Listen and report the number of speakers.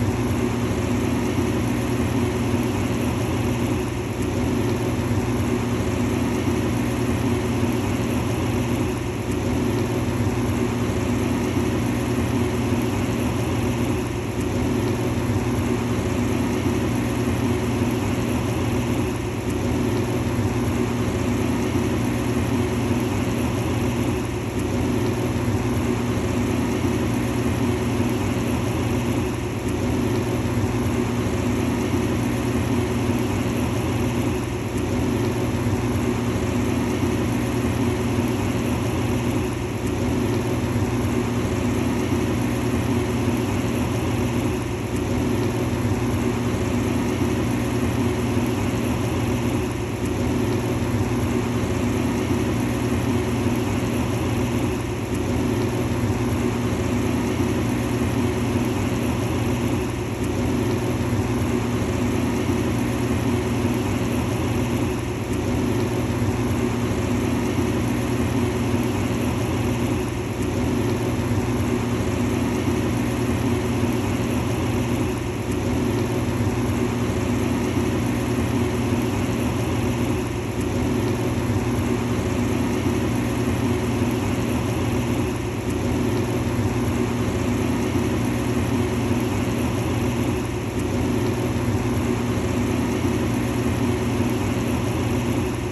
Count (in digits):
0